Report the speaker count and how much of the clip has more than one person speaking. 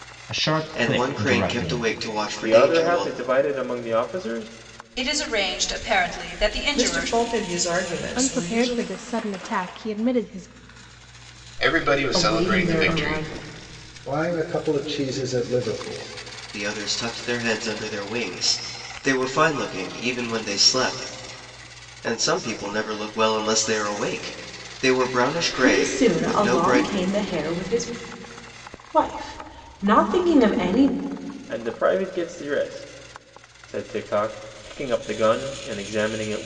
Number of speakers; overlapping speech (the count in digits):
9, about 16%